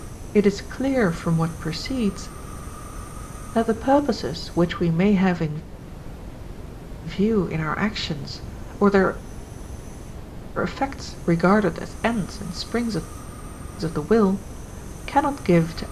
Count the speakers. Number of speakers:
1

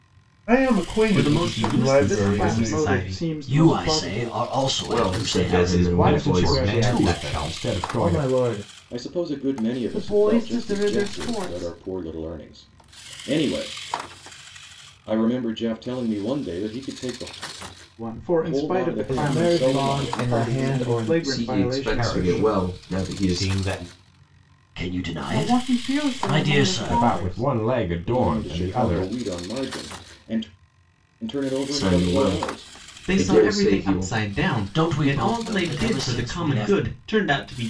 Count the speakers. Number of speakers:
10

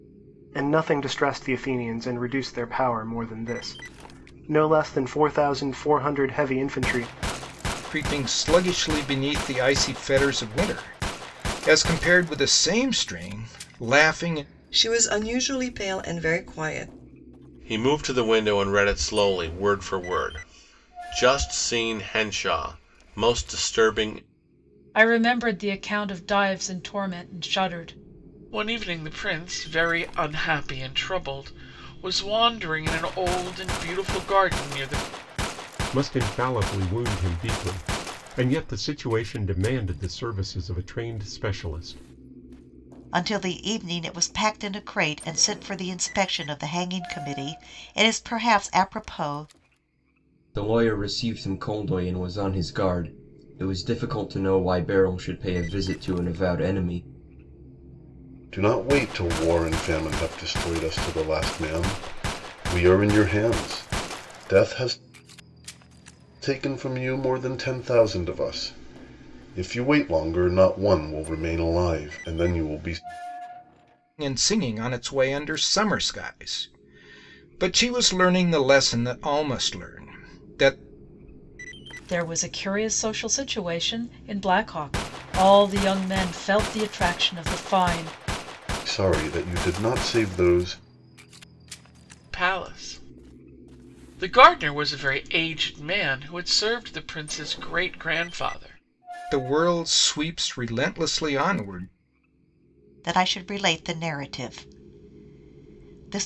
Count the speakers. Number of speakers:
10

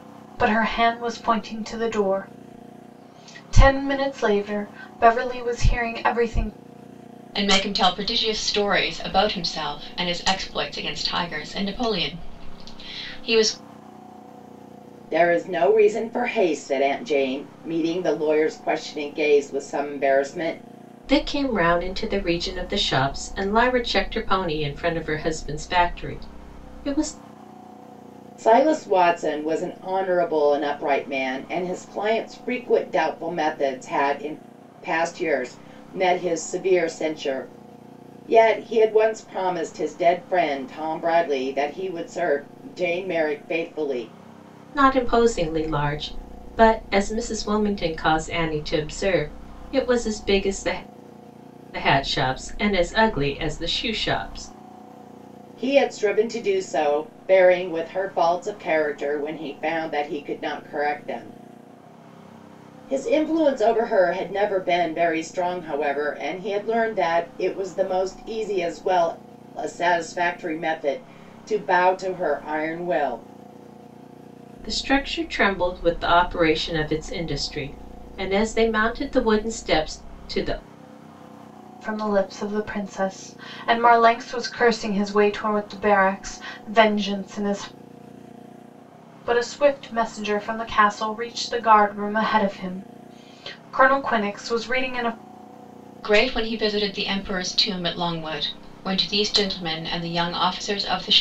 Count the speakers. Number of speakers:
4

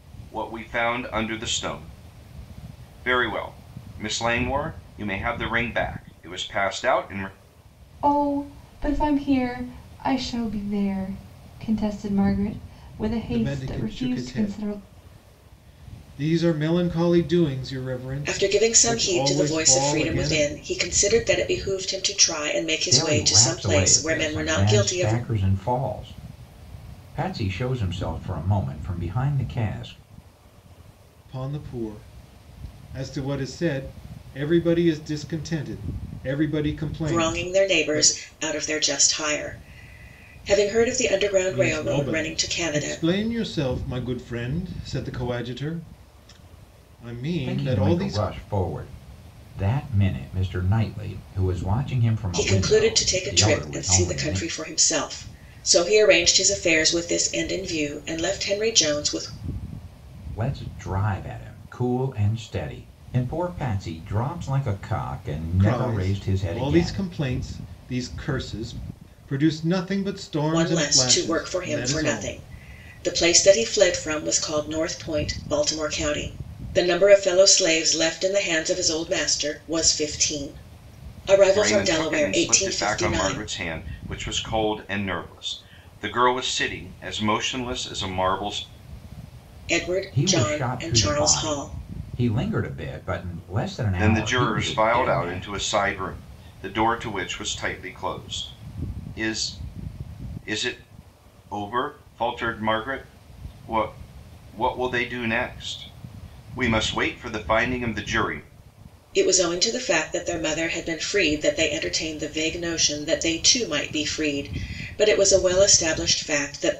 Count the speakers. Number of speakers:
5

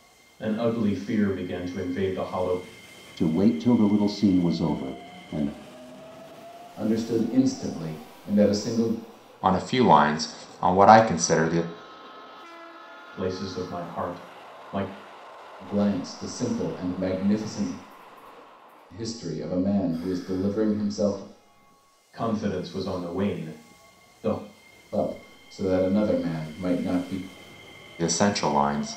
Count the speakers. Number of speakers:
4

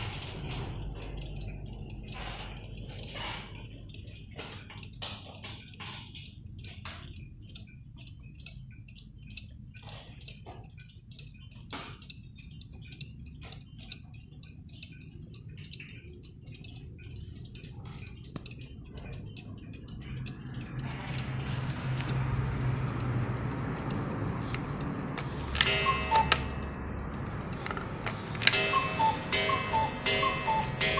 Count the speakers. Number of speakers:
0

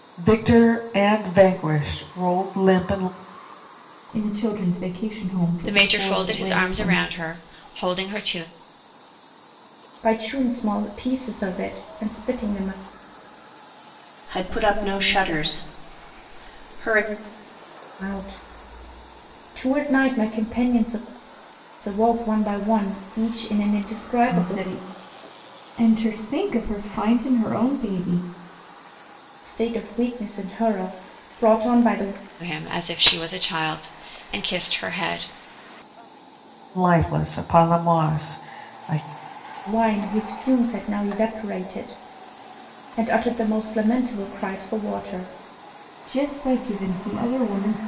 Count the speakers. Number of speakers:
5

